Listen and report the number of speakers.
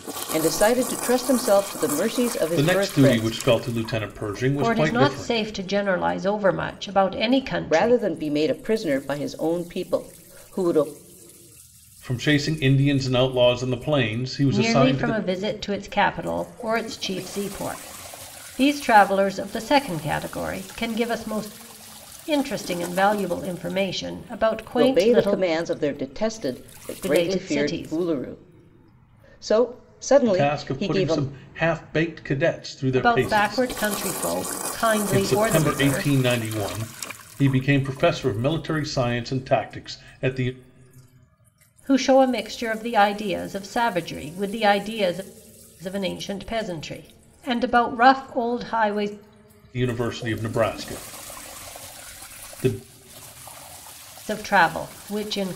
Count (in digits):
3